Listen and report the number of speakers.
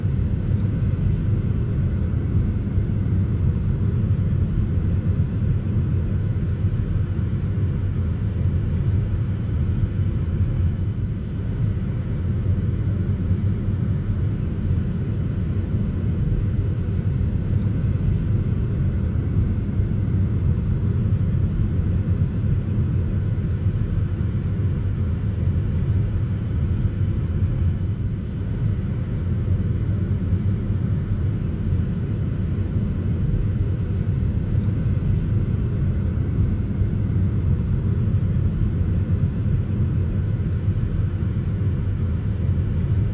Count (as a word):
zero